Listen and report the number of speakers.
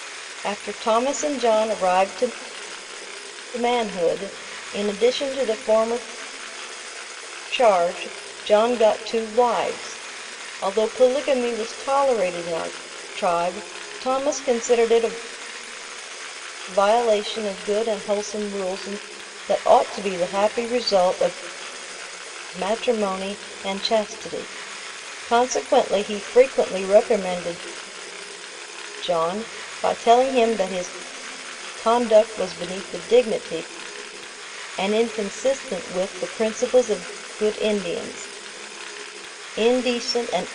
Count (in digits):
1